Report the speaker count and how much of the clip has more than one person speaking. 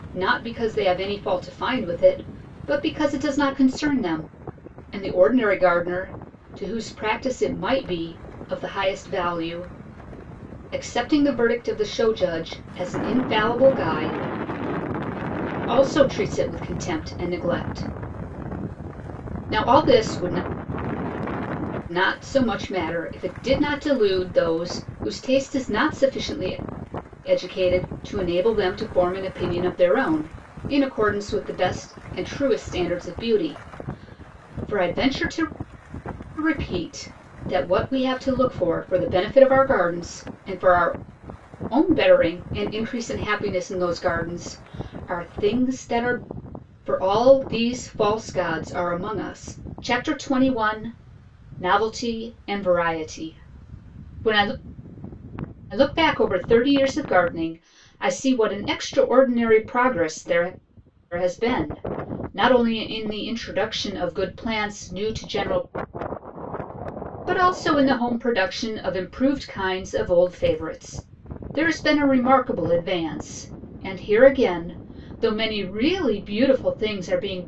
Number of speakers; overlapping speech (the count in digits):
1, no overlap